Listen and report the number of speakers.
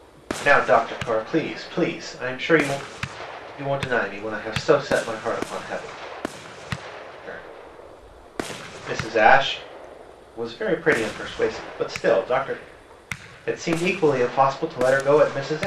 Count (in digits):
1